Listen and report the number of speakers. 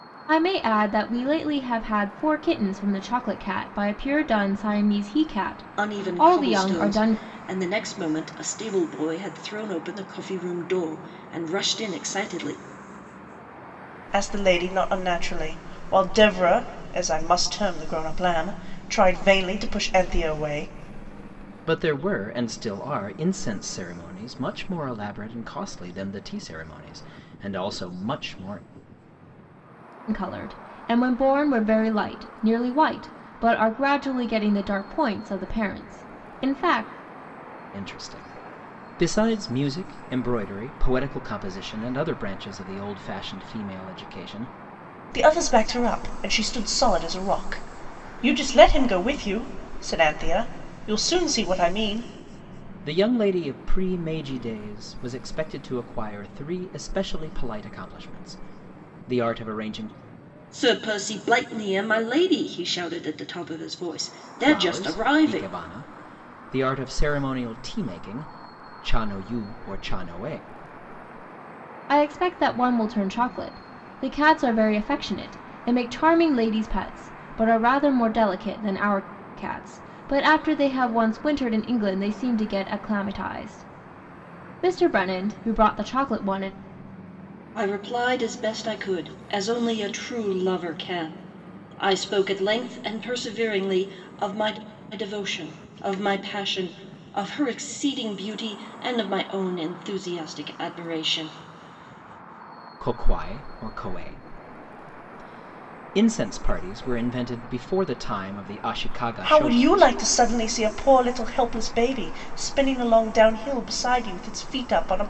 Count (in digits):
4